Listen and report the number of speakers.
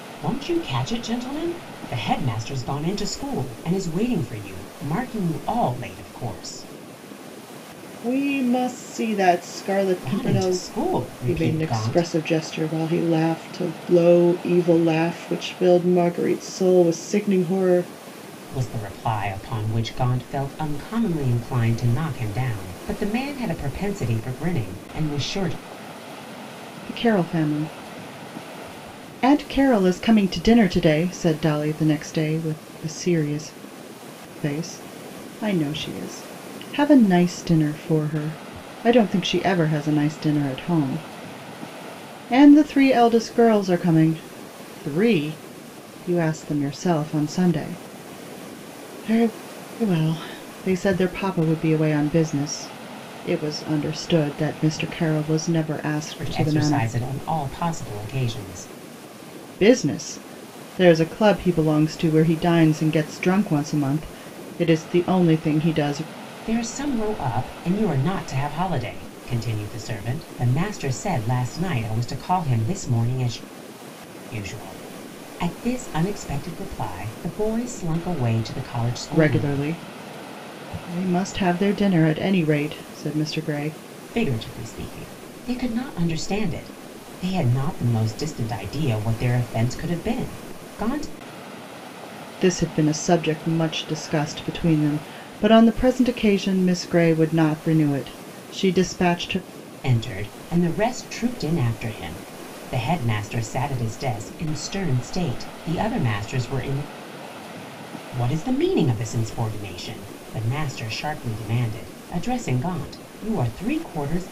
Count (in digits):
2